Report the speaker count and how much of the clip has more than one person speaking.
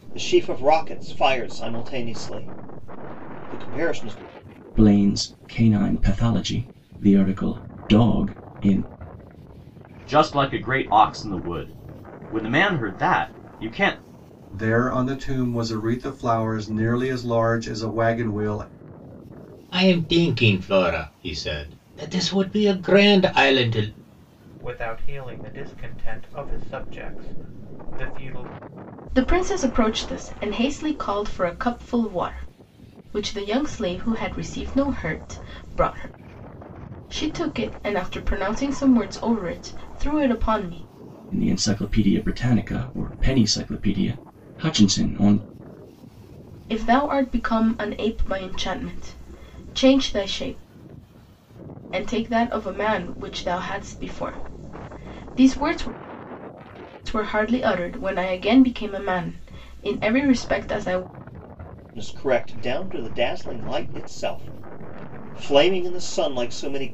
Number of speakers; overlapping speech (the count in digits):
7, no overlap